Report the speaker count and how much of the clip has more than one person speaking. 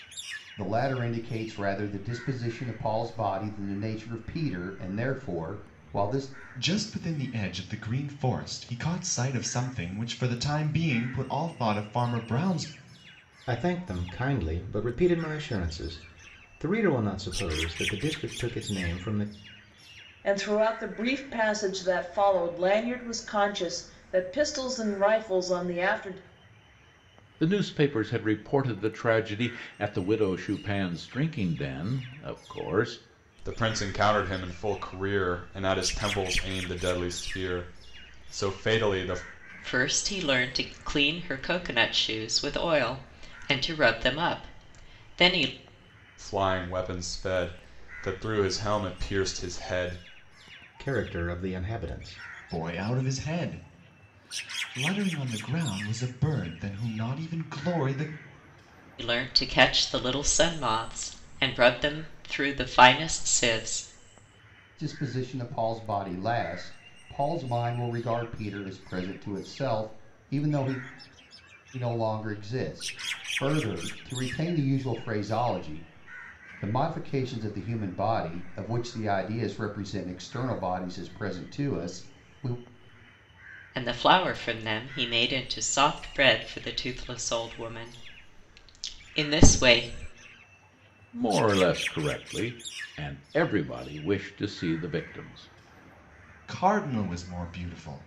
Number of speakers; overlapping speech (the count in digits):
7, no overlap